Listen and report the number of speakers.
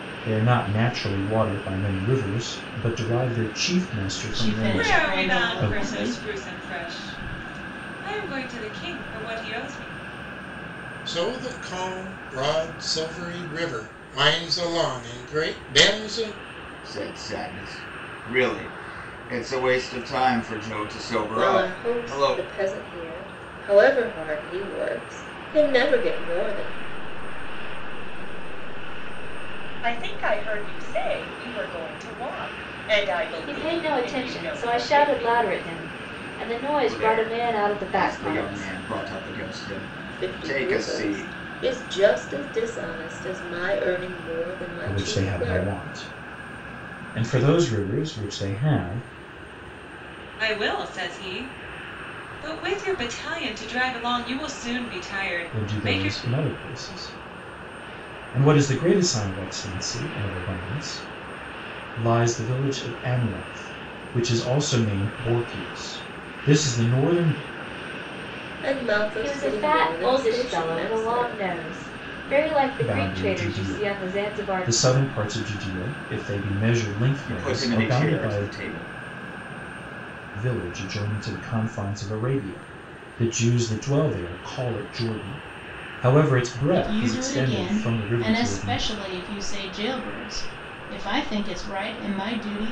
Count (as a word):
nine